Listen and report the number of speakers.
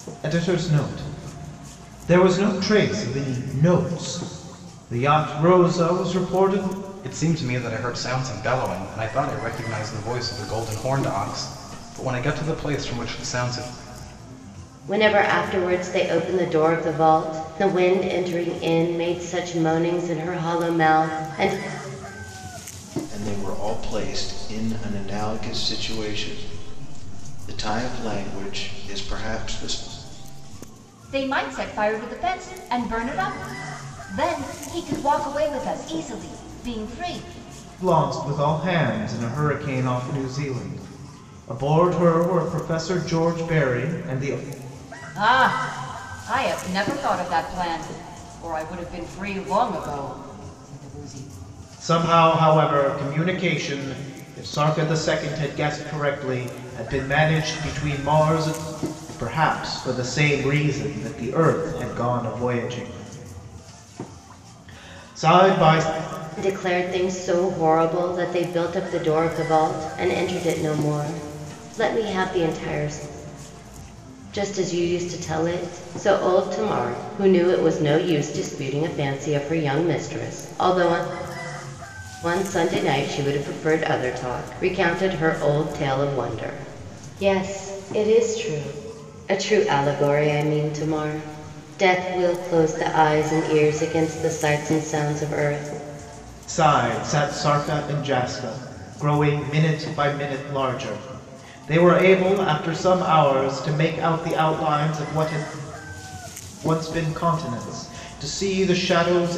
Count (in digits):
5